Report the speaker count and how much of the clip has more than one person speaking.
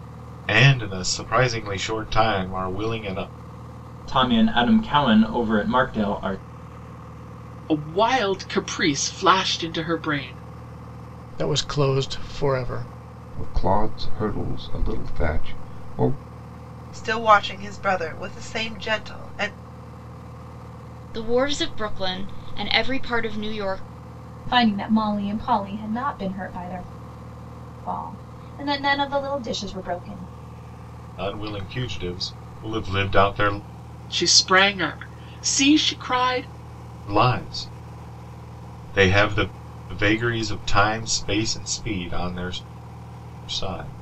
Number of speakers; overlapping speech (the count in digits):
8, no overlap